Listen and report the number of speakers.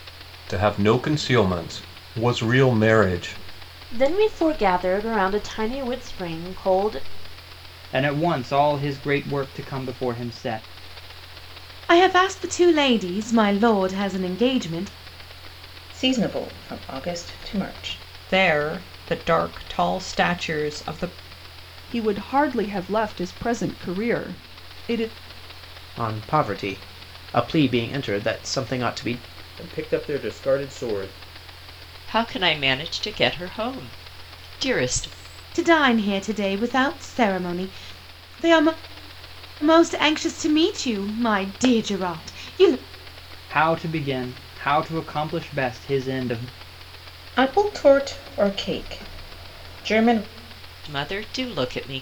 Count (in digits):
10